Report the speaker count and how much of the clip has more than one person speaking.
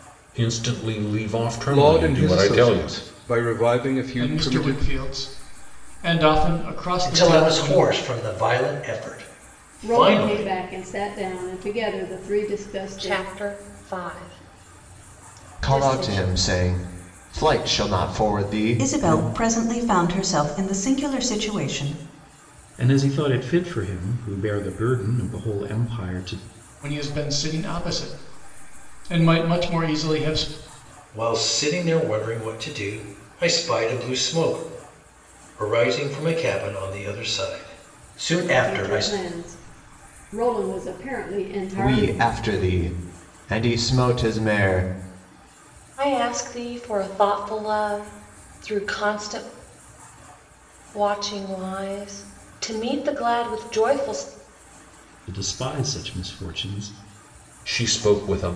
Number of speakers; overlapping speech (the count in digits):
9, about 10%